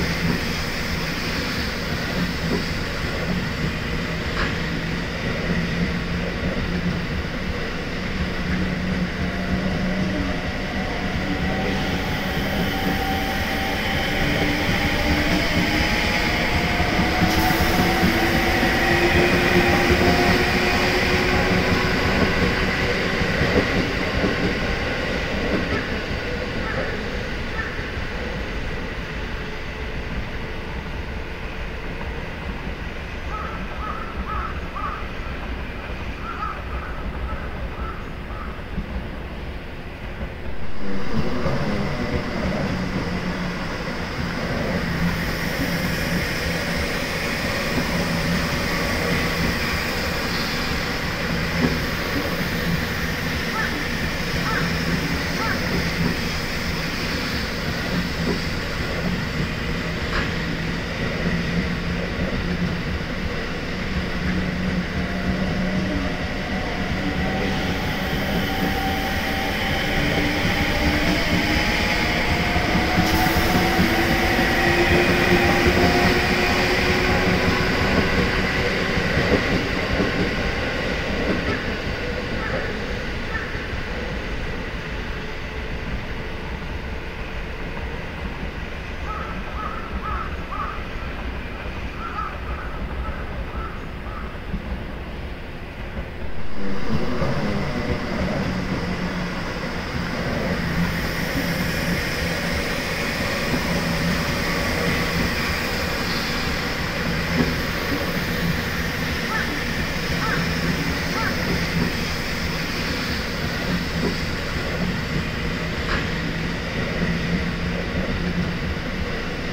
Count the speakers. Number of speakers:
0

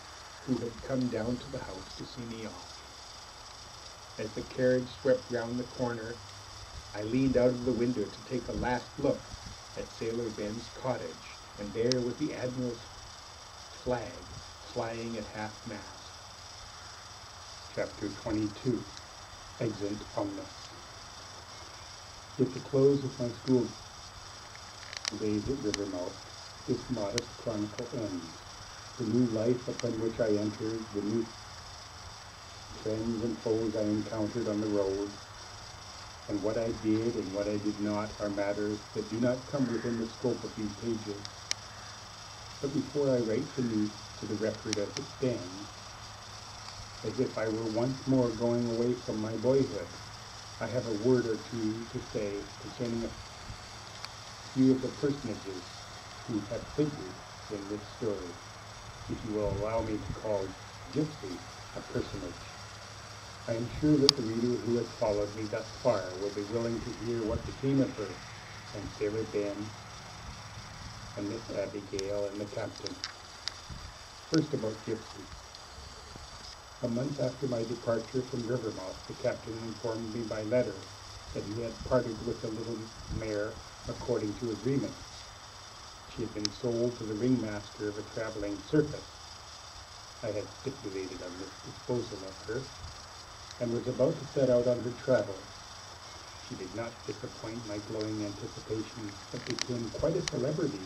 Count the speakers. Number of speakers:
1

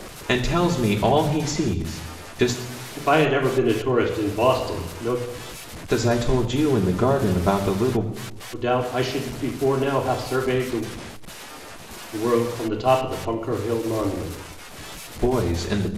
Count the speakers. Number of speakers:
2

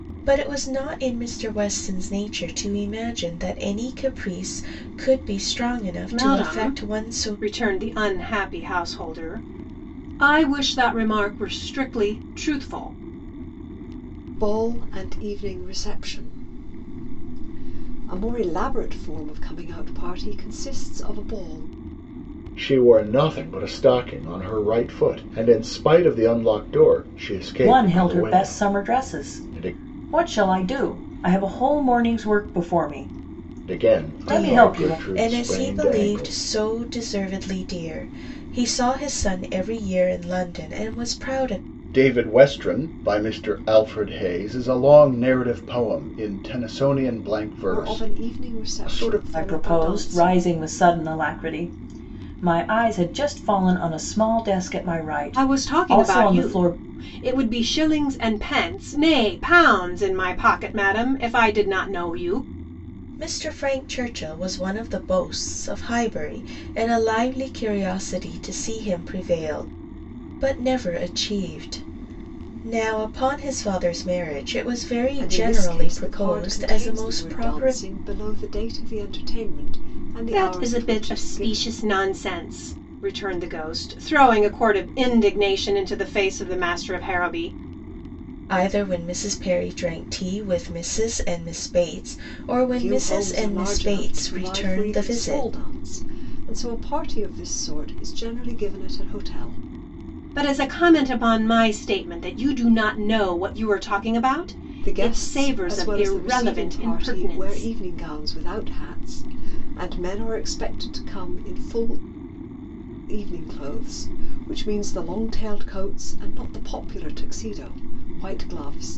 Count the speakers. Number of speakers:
5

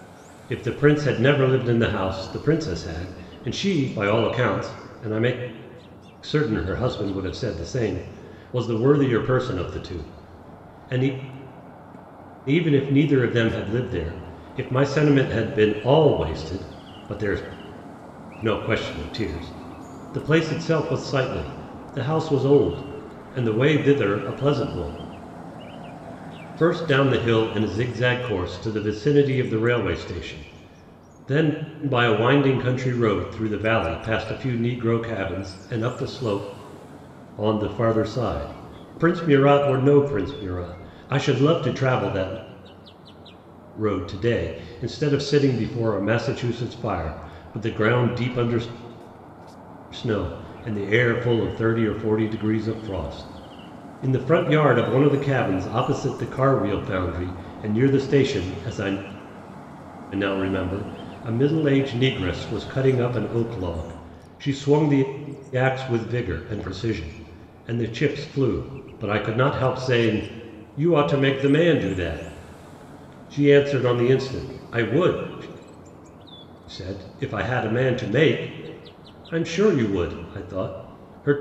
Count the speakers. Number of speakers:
1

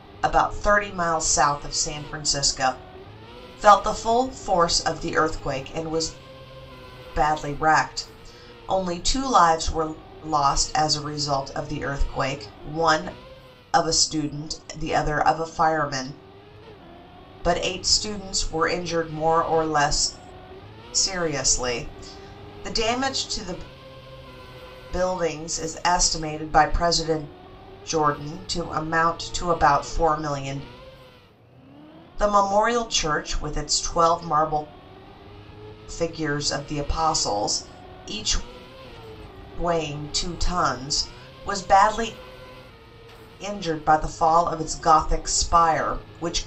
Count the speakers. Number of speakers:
1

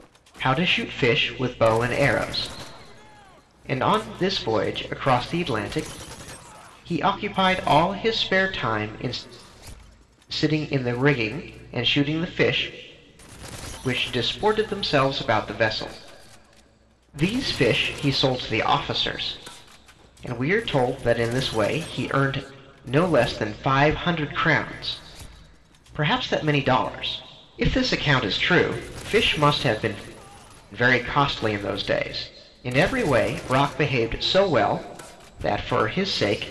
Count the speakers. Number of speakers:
1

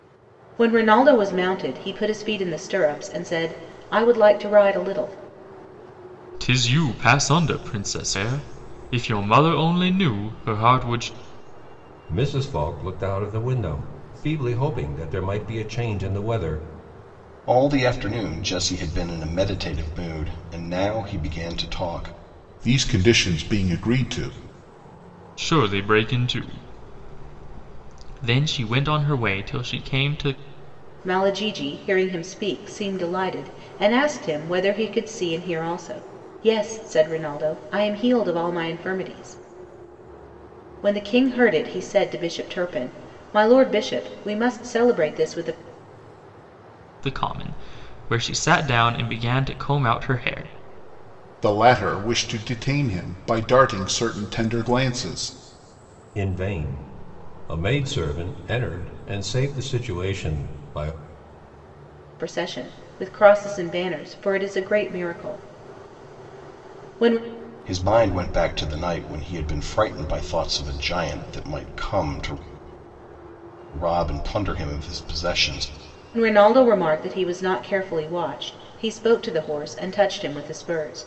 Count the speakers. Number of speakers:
5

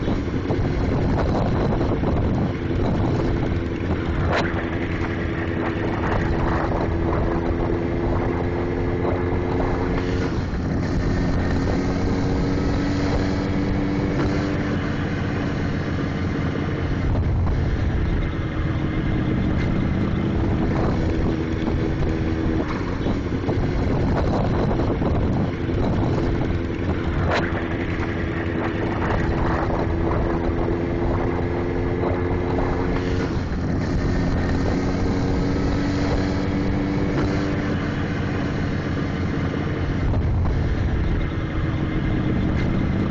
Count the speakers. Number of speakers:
0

